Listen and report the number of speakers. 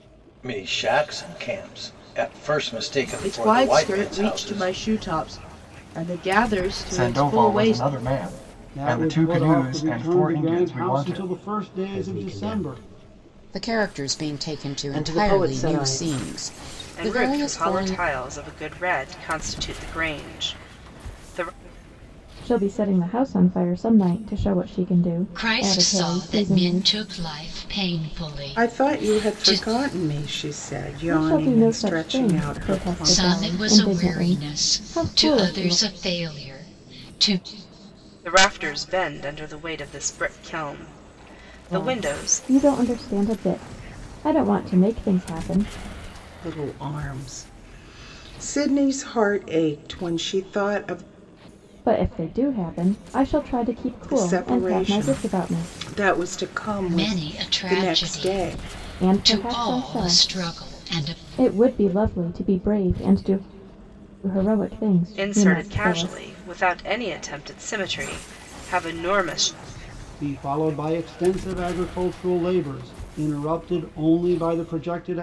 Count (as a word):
ten